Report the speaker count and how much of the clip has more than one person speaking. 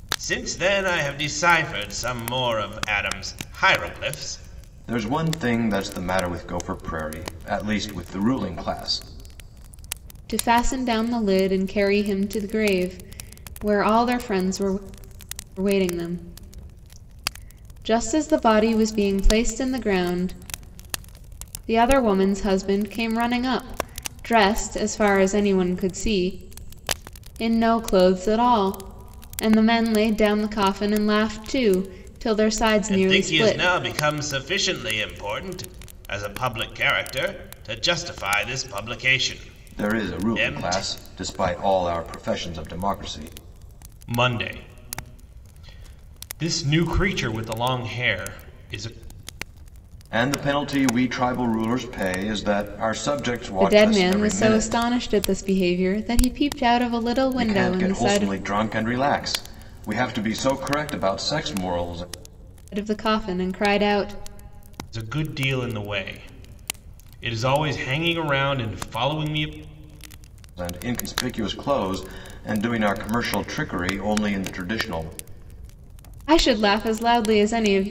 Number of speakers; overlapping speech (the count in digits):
3, about 6%